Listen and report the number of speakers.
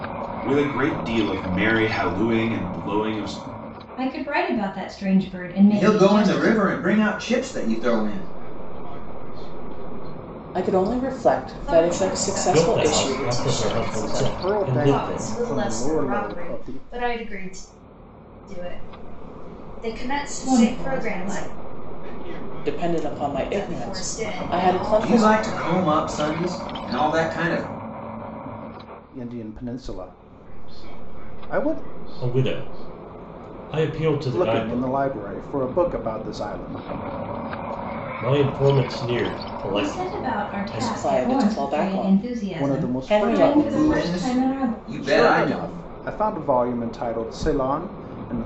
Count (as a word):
eight